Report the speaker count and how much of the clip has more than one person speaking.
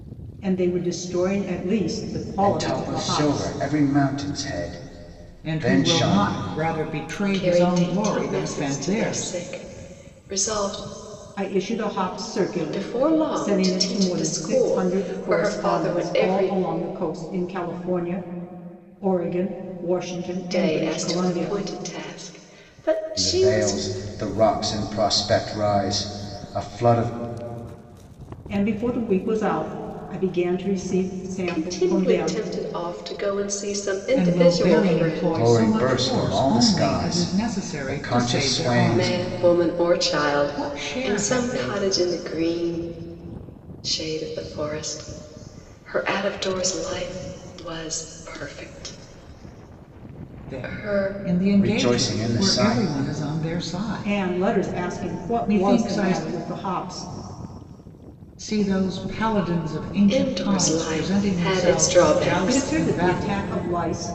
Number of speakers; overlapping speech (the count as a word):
four, about 41%